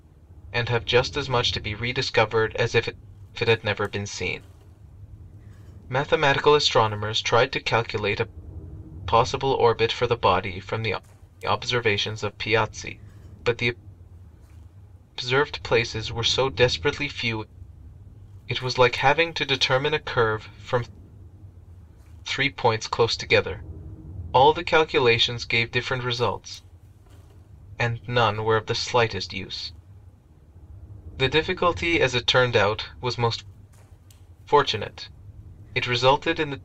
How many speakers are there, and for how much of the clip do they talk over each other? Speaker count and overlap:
1, no overlap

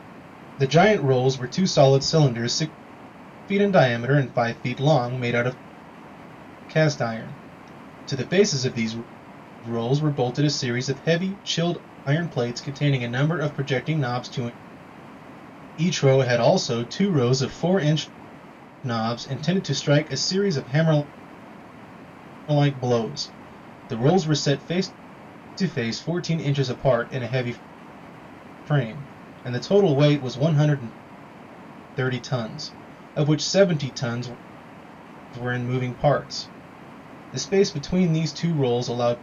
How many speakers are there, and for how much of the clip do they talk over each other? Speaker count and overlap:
1, no overlap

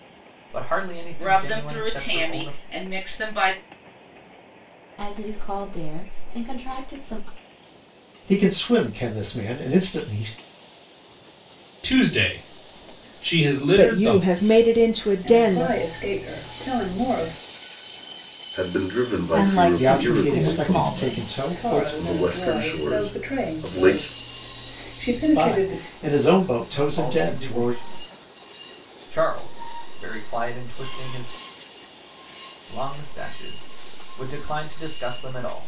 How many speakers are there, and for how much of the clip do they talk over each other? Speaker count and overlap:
9, about 25%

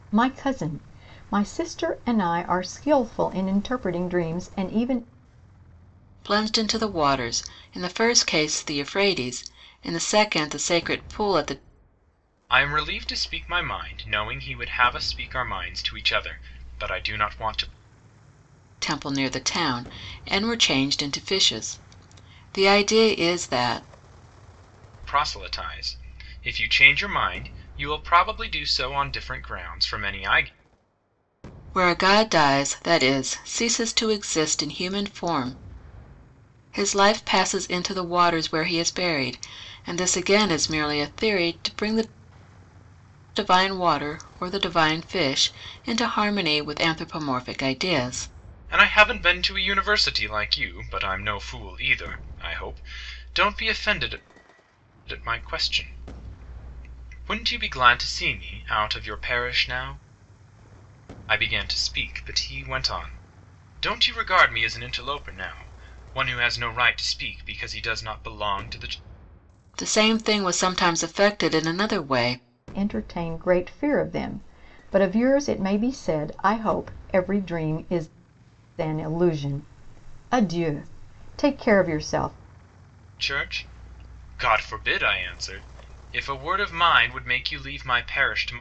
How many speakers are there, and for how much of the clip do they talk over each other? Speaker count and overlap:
3, no overlap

